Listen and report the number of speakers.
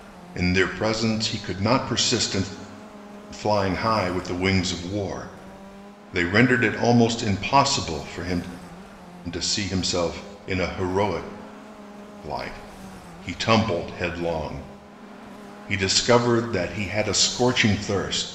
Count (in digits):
1